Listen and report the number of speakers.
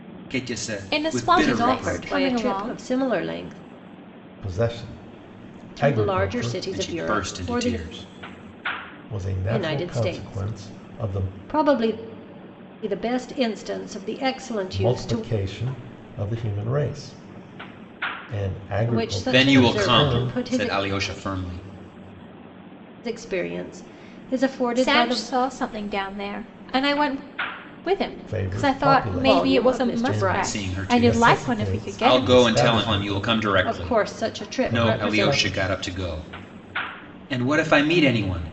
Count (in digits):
4